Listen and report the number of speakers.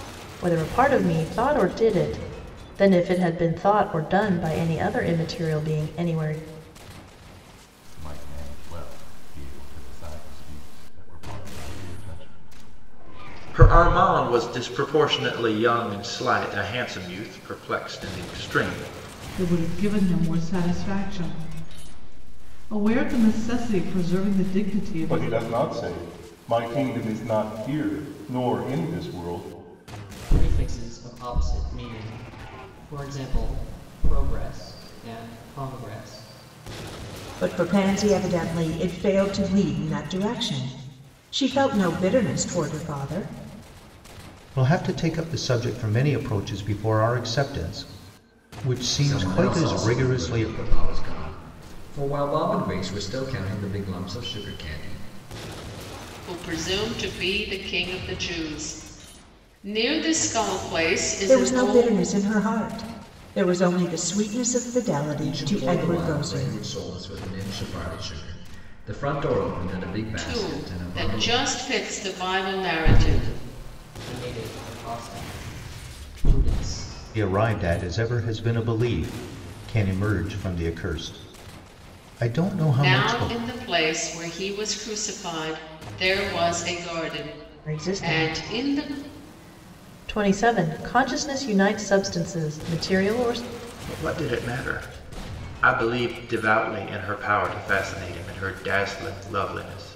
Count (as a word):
ten